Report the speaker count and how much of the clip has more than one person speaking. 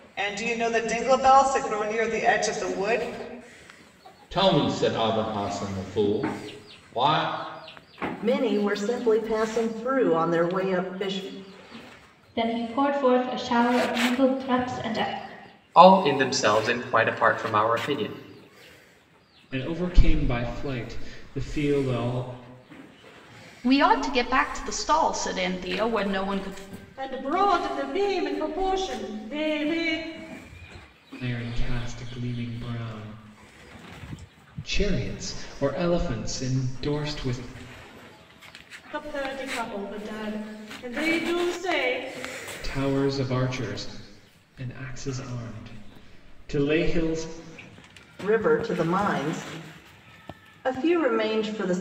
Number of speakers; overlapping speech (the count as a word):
eight, no overlap